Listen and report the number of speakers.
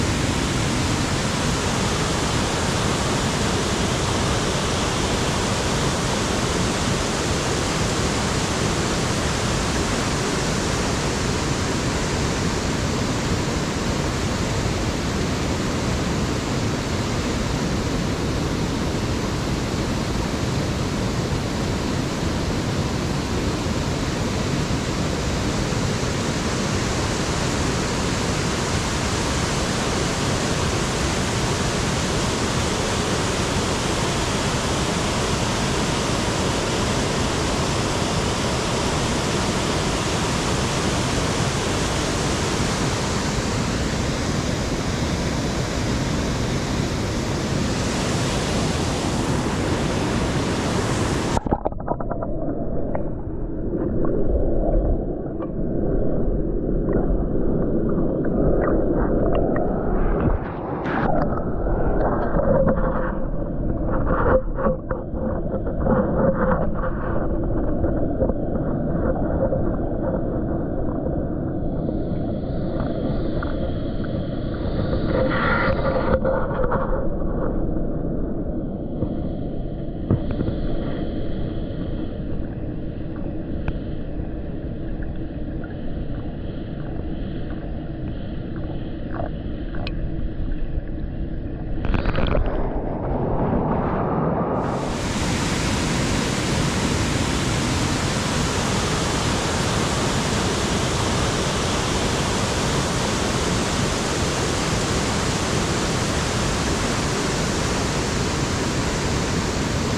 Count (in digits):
0